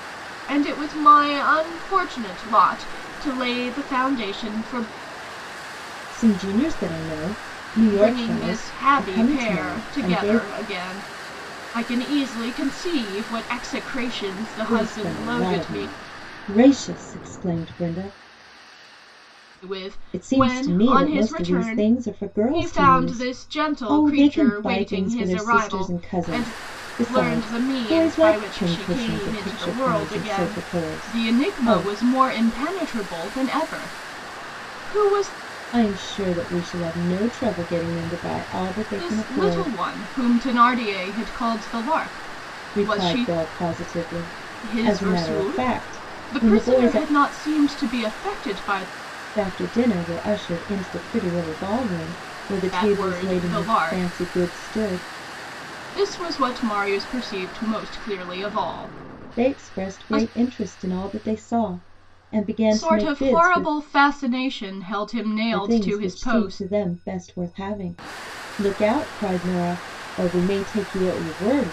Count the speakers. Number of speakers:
2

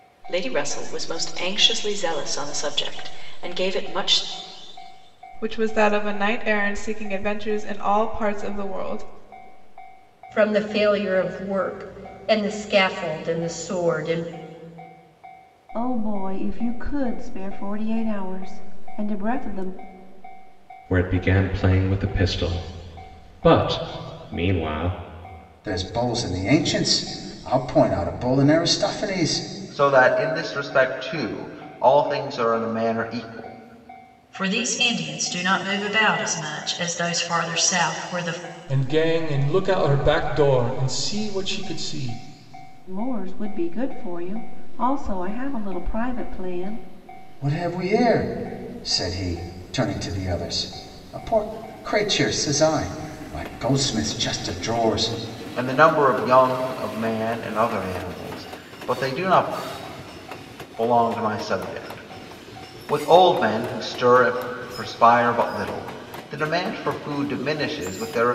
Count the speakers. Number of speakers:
9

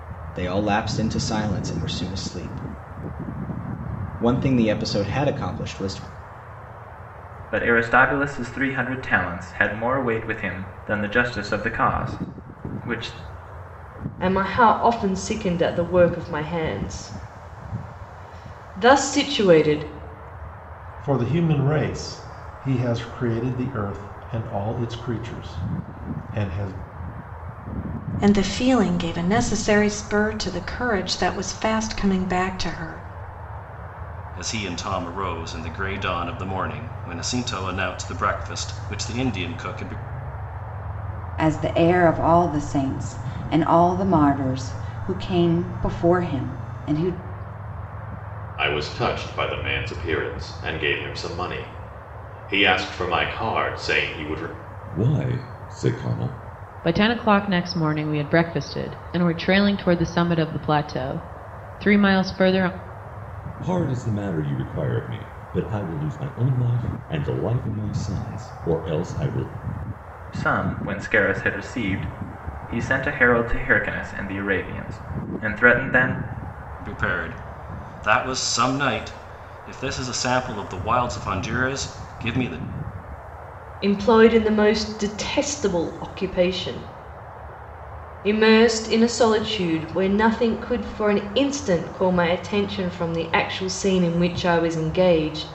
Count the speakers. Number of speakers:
10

